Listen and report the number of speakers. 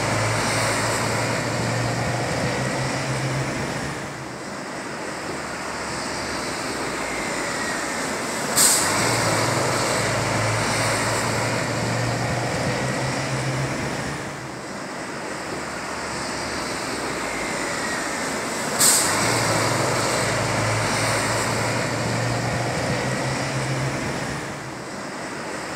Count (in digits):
0